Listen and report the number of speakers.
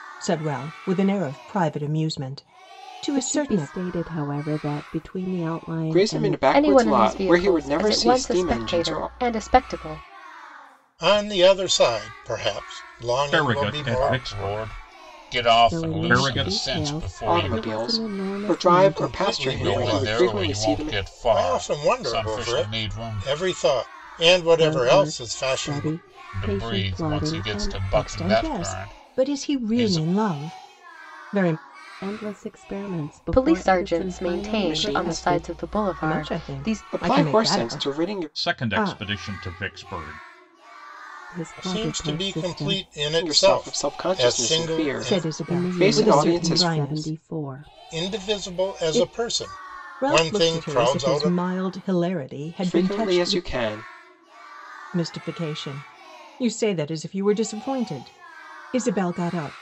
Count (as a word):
seven